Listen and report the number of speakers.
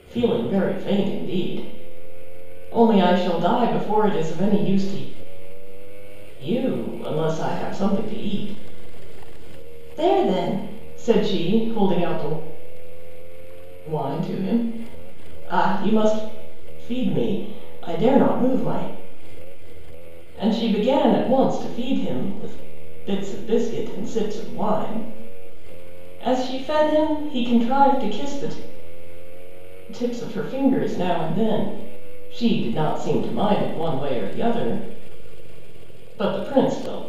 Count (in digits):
1